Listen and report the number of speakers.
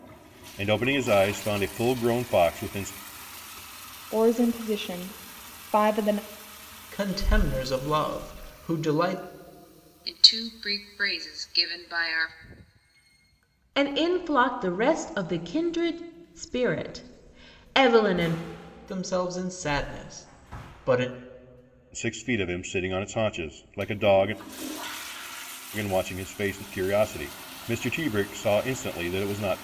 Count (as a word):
five